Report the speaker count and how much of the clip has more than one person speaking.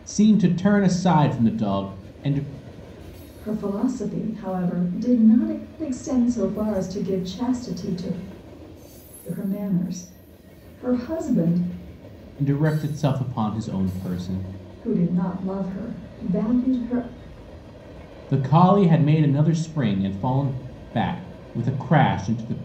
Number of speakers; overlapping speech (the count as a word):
two, no overlap